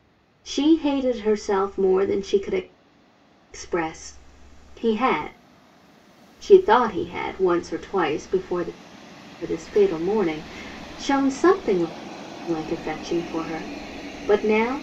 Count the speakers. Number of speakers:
one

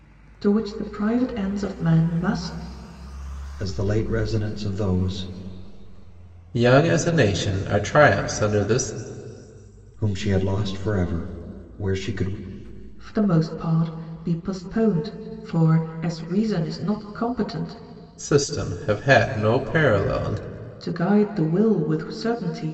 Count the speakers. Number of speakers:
three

